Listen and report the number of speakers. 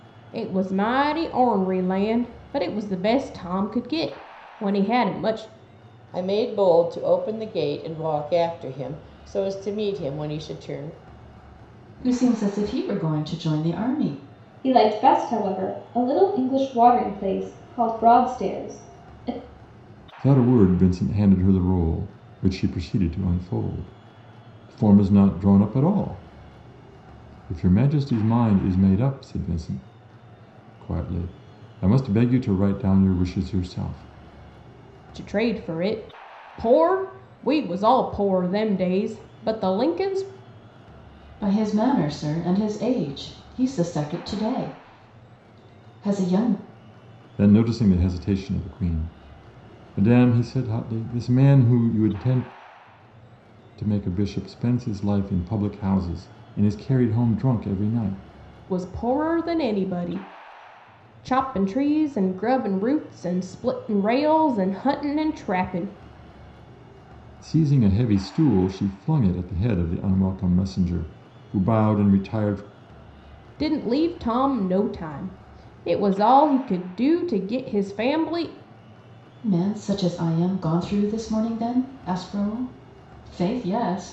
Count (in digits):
5